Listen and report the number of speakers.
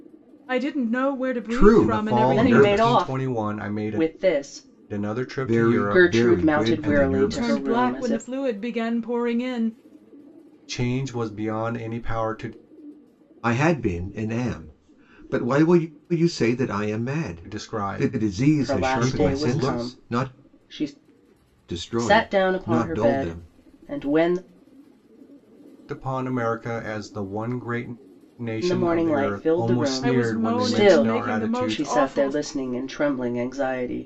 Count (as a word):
four